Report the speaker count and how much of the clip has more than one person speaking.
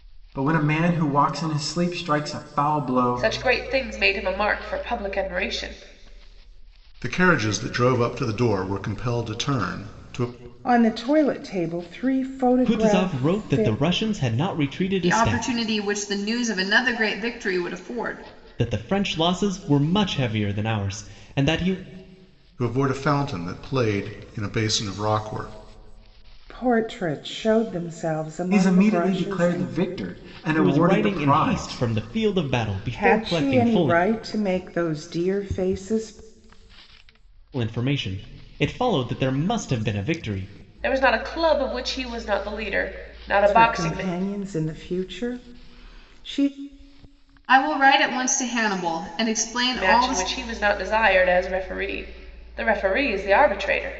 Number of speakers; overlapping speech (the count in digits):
6, about 13%